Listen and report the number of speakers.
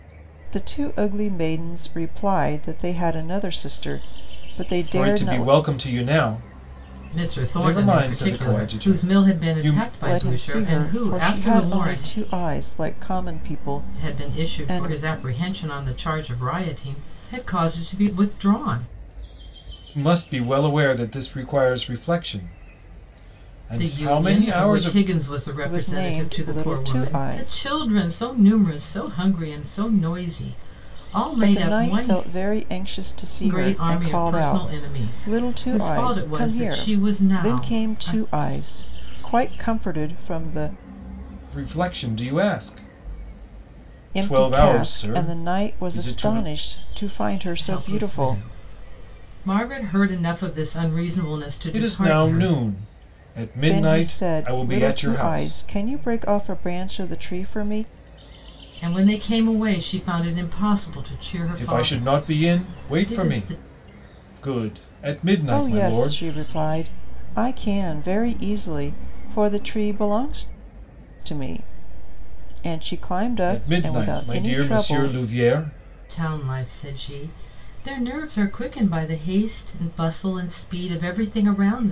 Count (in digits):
3